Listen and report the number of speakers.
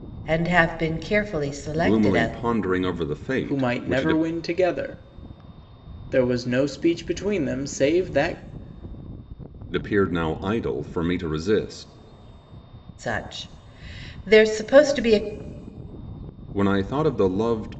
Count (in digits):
3